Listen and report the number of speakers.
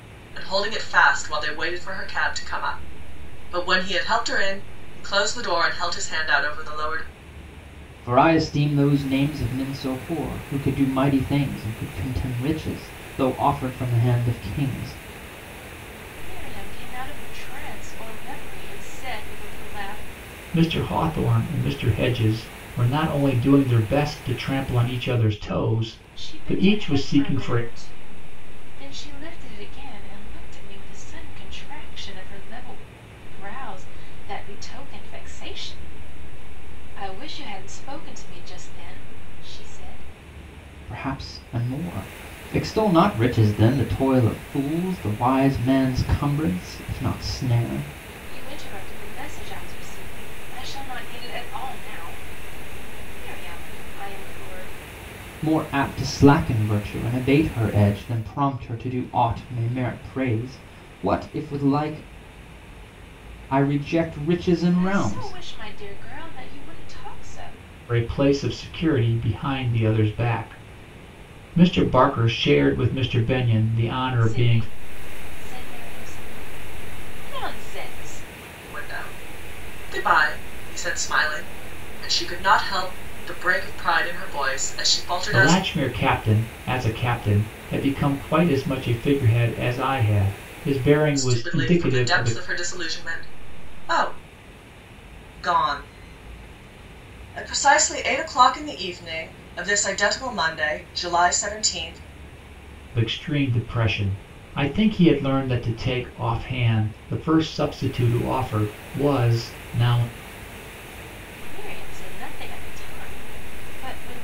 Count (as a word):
four